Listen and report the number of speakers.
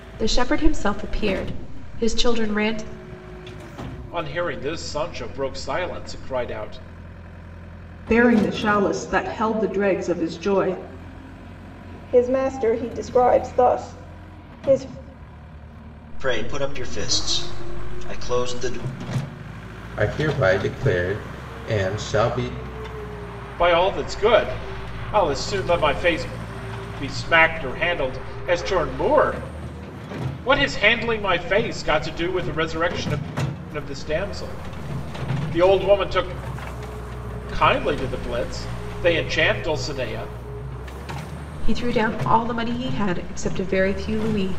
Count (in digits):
6